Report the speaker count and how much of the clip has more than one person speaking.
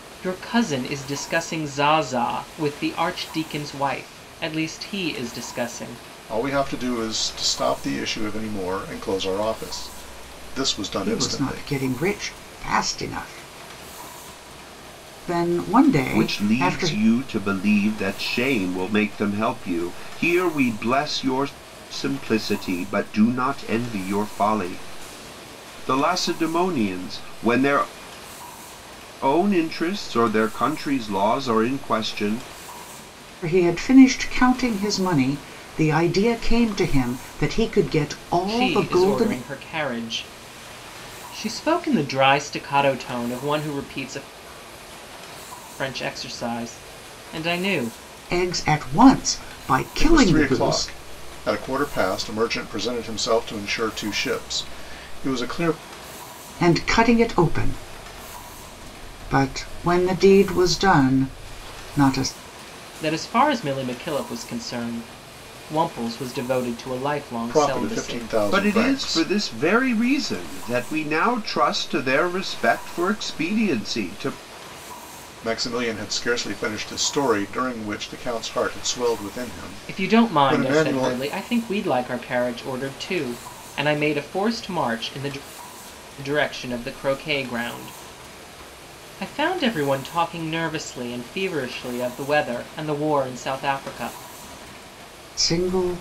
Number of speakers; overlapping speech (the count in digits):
4, about 7%